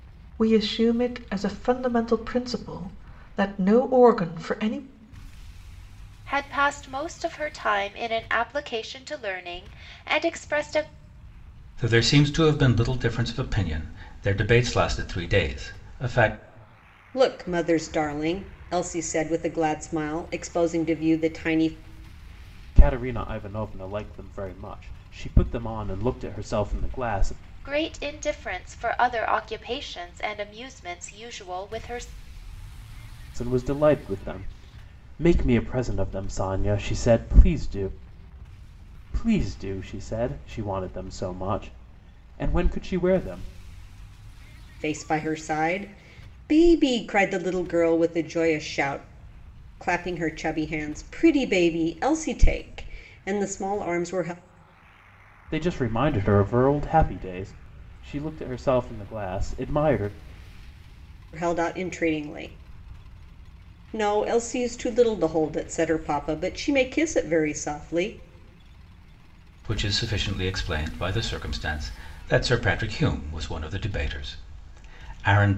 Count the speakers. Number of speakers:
5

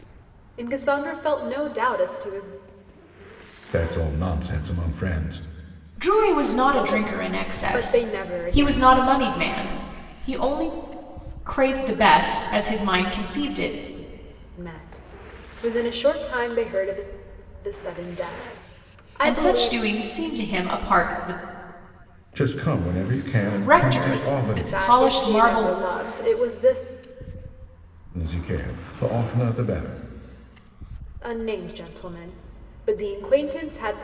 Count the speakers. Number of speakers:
3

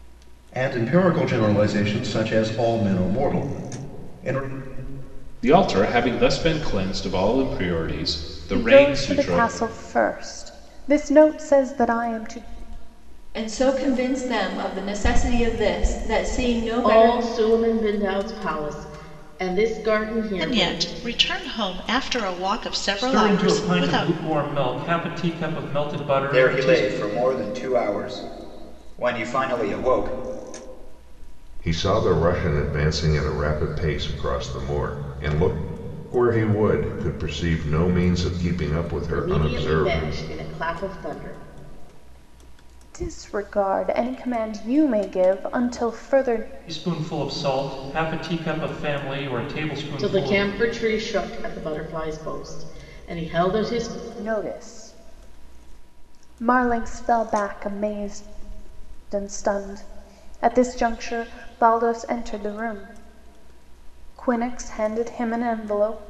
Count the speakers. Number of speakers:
9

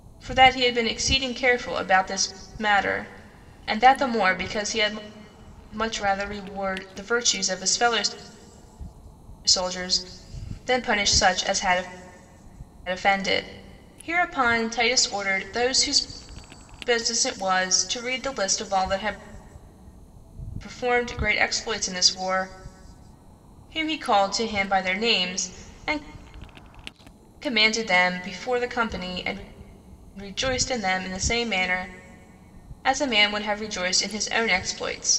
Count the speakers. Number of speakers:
1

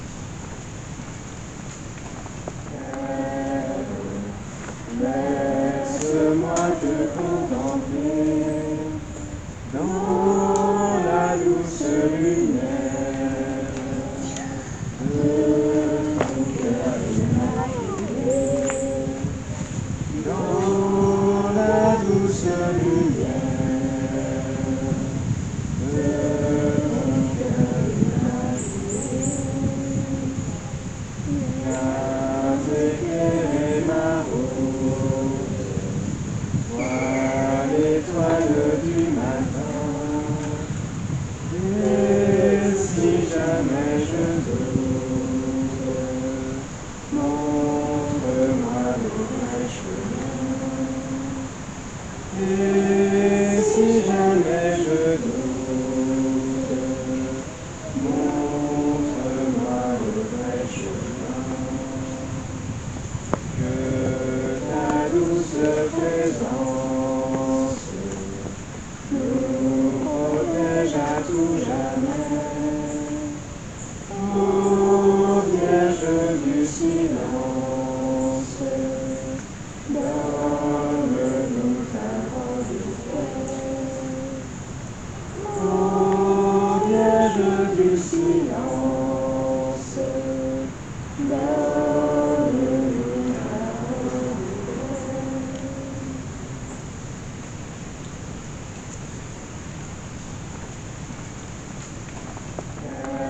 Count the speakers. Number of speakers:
0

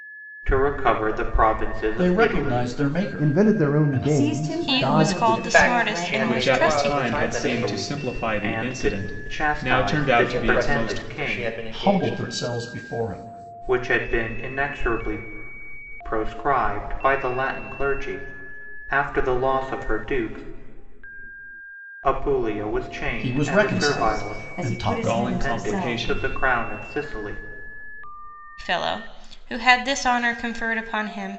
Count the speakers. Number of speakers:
7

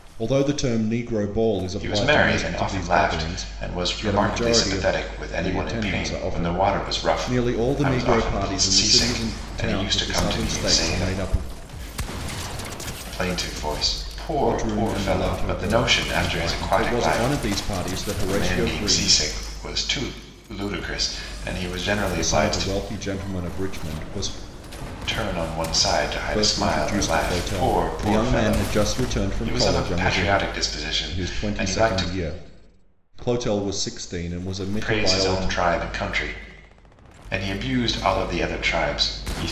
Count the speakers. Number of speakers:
2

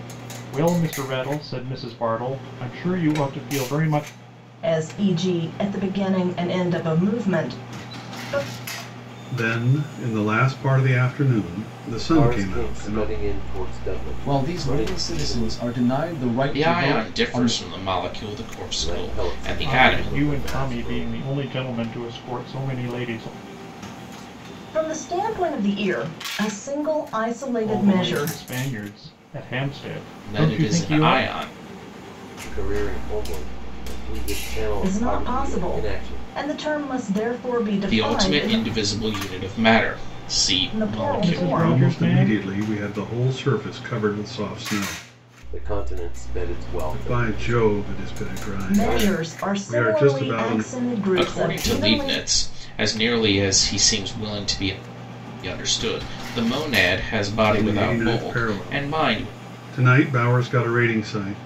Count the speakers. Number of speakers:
6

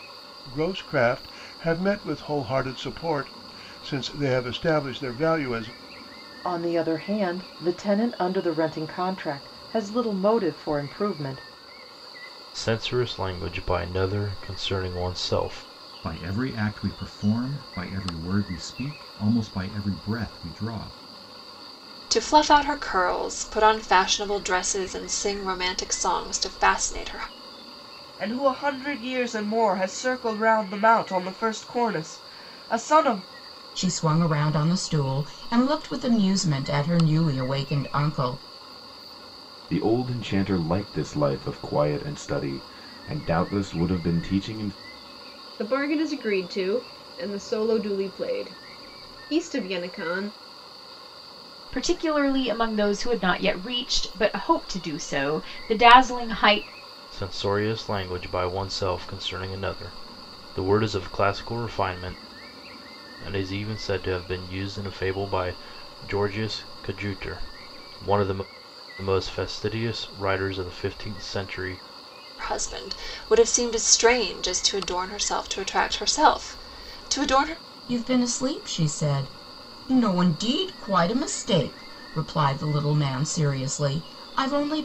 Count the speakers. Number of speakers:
10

